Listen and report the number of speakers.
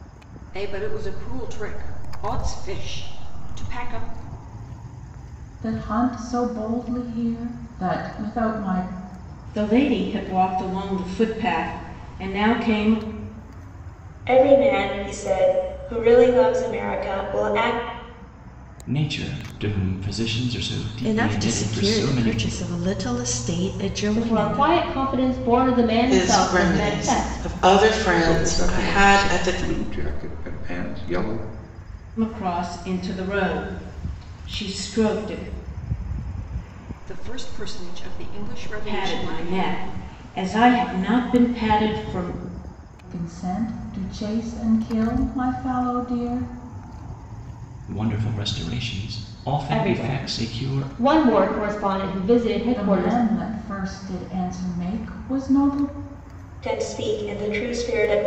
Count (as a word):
nine